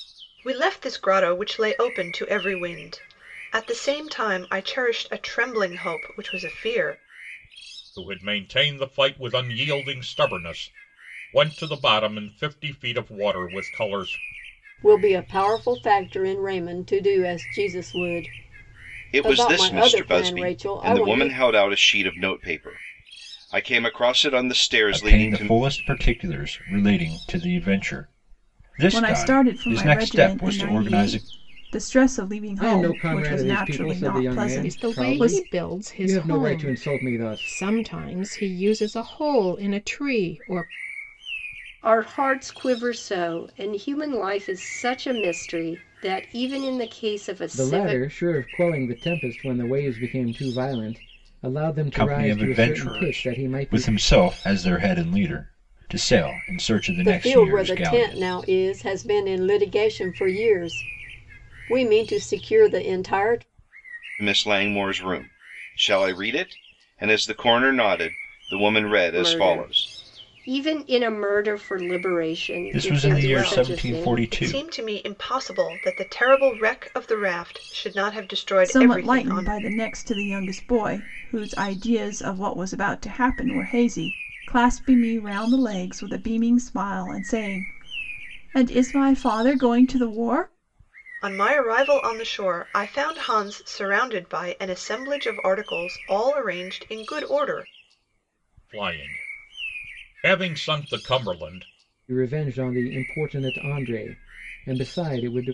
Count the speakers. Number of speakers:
9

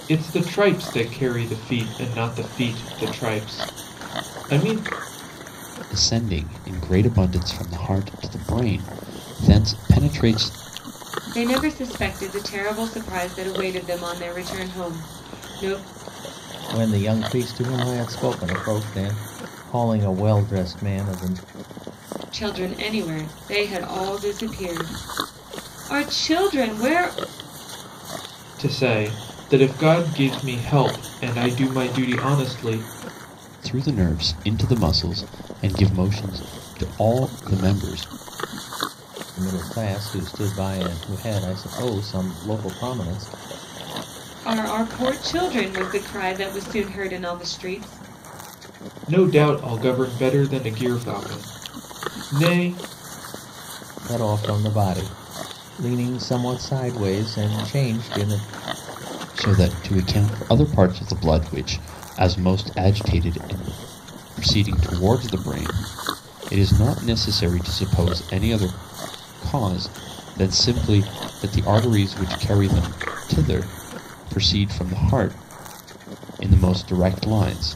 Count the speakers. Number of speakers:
4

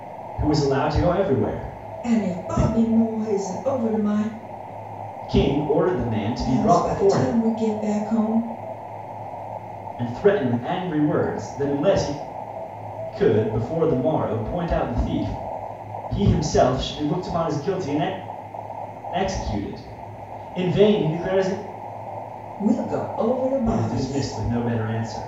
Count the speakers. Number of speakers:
2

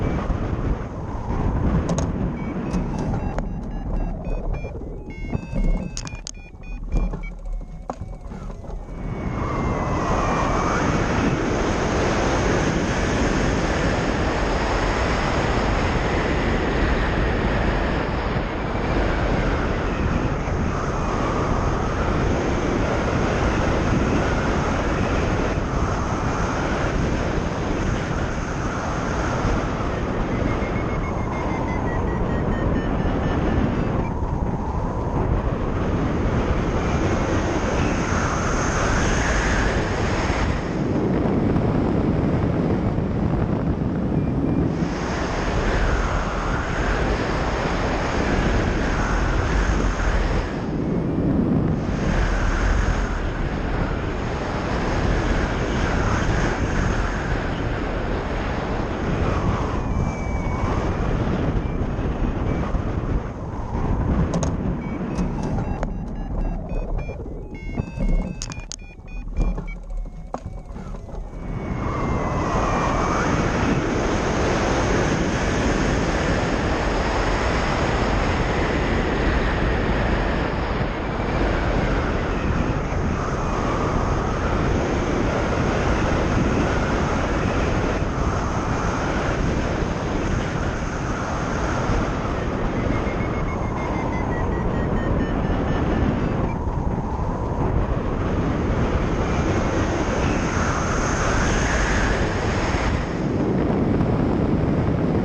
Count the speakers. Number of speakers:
0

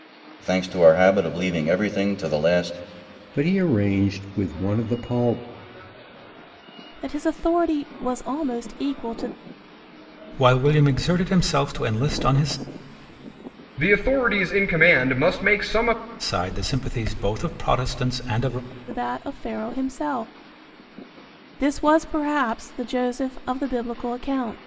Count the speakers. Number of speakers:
5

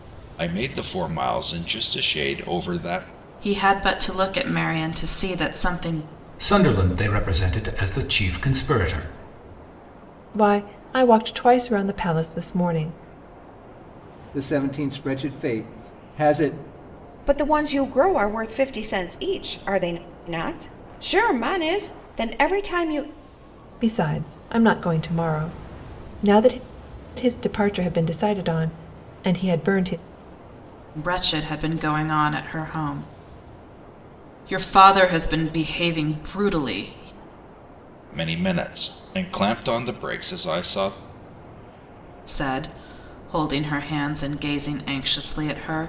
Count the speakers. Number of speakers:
6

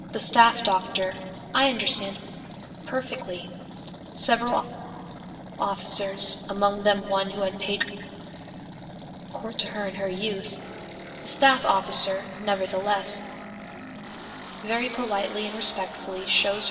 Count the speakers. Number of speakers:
1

